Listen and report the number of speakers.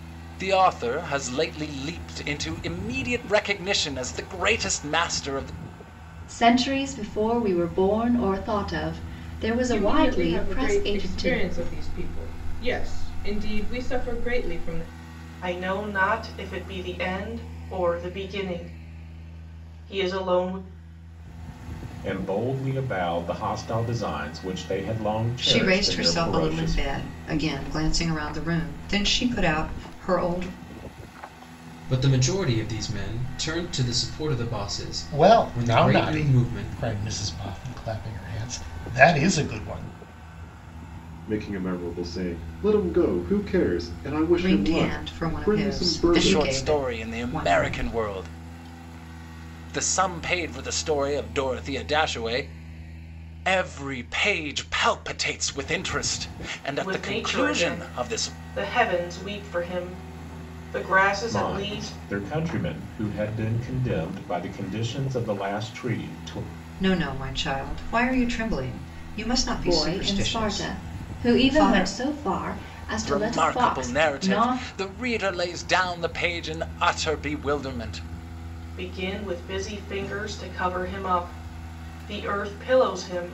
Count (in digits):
9